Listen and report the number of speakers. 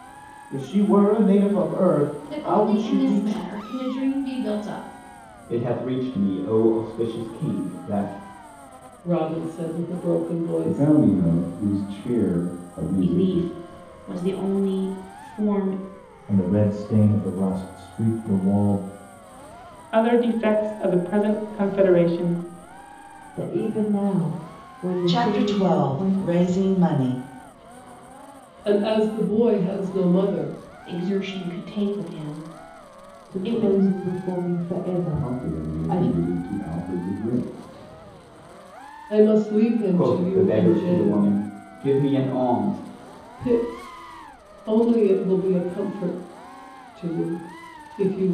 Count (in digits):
10